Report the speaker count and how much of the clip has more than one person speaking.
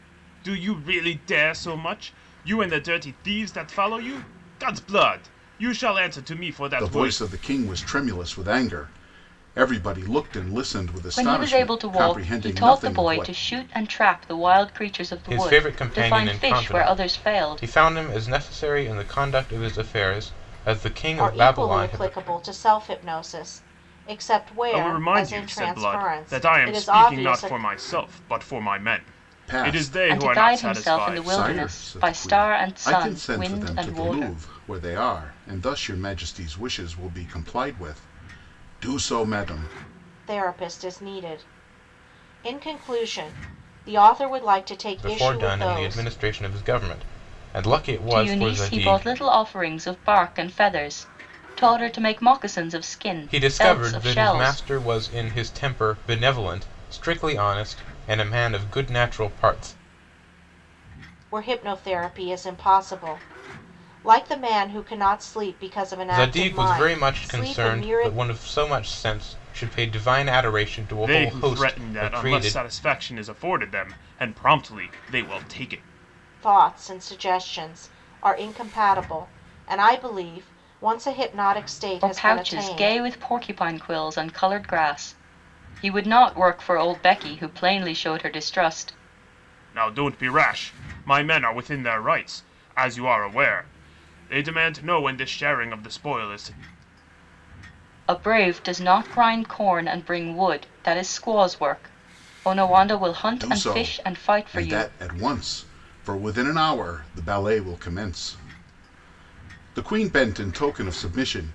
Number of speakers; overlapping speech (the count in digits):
5, about 21%